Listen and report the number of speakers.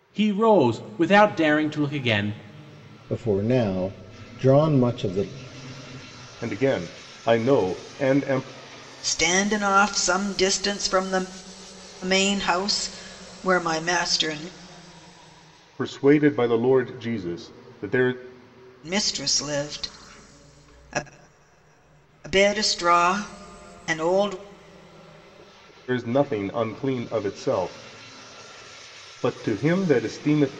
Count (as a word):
four